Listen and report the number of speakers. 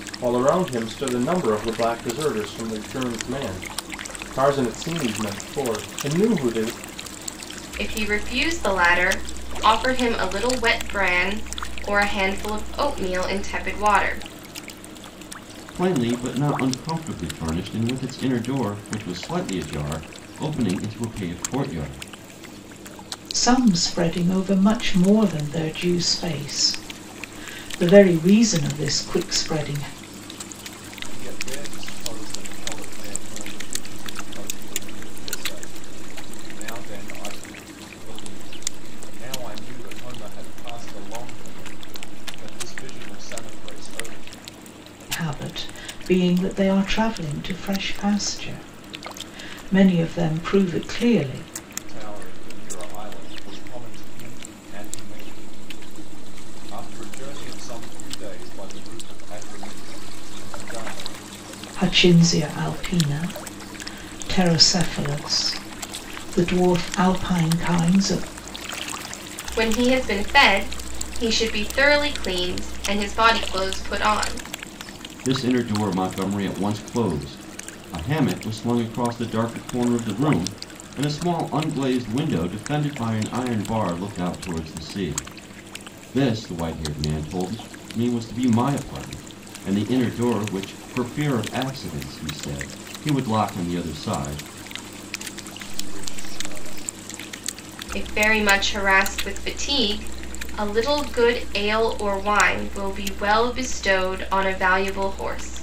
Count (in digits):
5